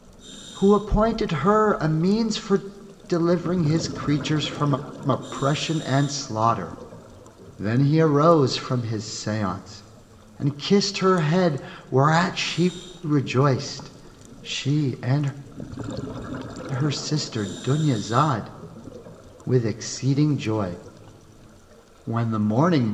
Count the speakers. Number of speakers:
1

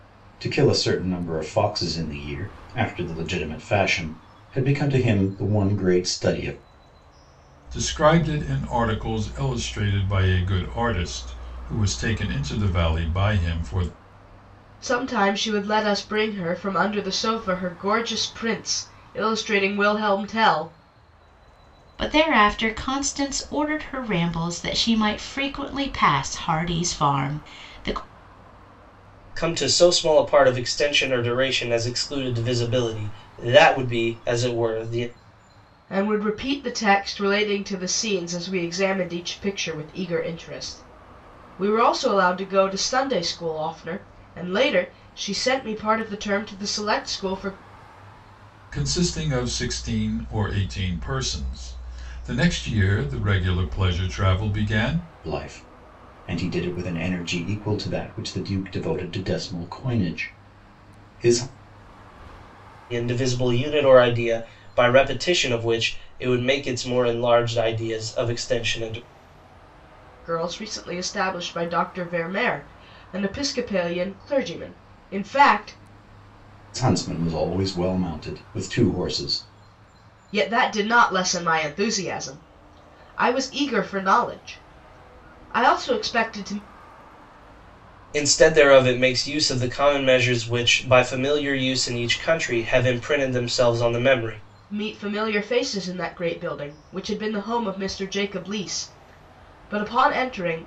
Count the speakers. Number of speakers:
5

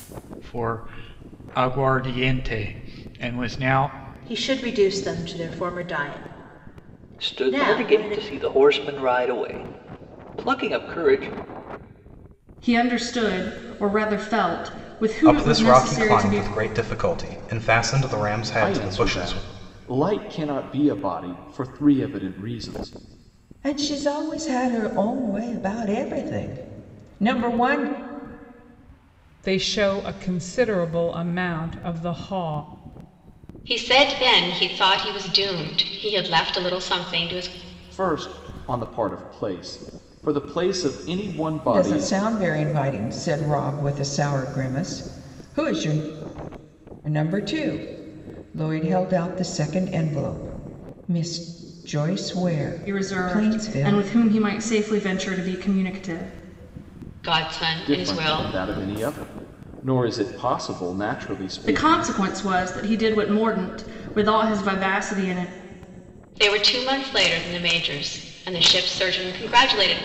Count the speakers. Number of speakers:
9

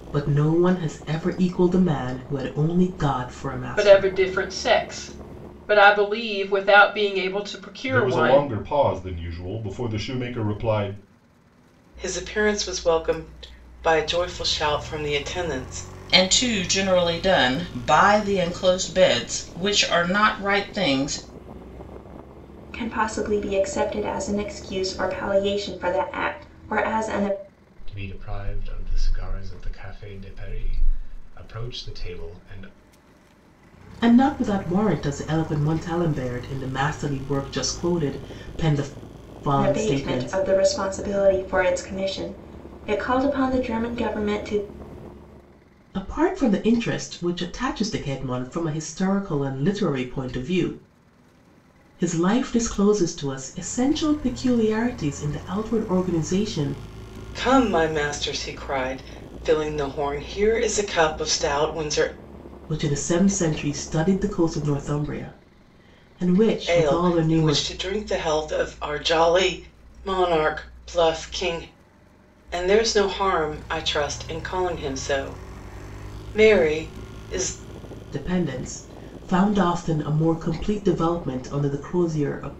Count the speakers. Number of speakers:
7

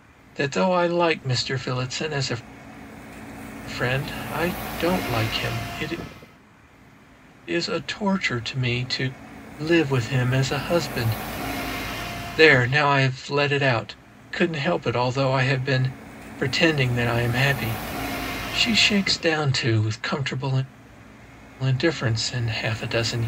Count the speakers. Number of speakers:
1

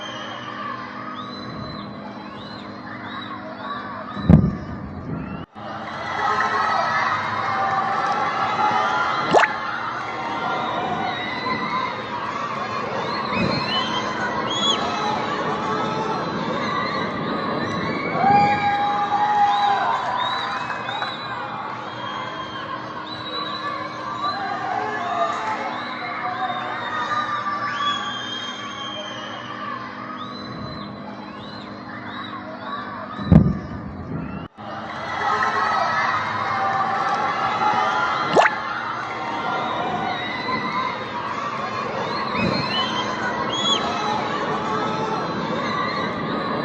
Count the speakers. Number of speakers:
0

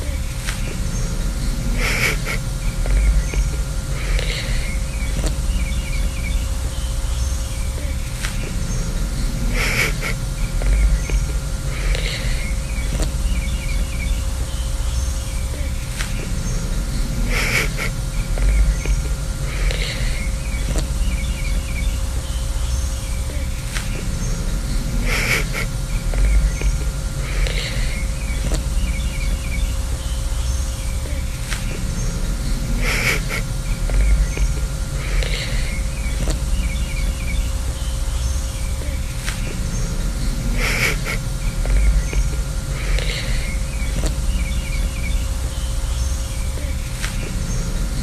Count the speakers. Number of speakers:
0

